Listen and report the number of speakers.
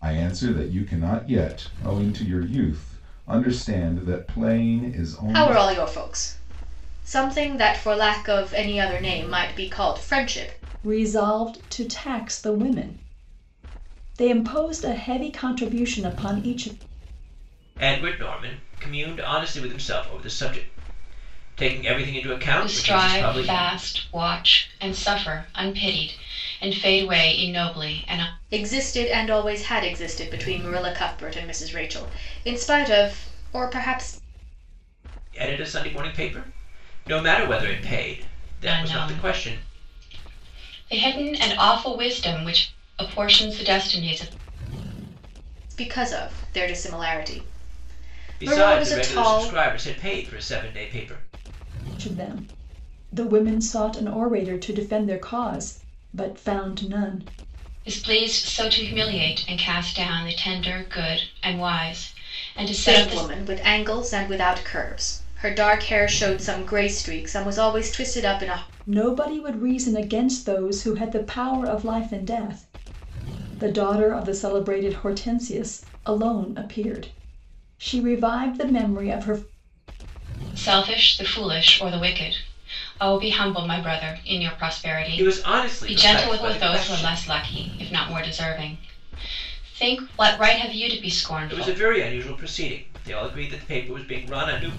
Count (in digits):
5